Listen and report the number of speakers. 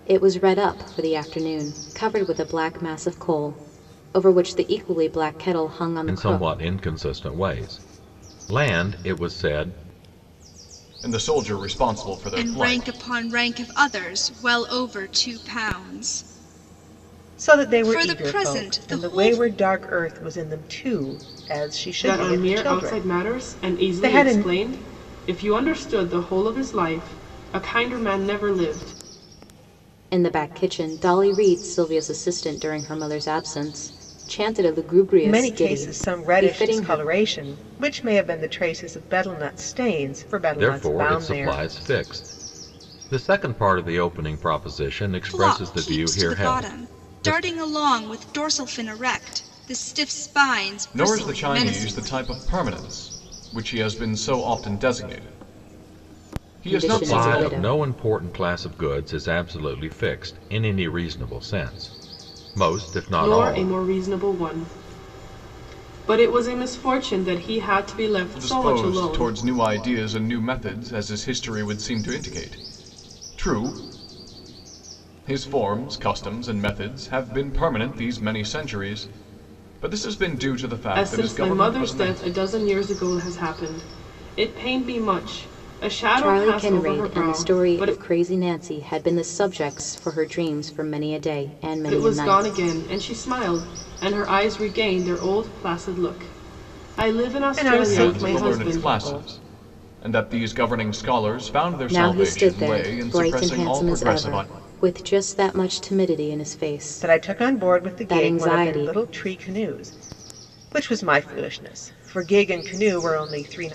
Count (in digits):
6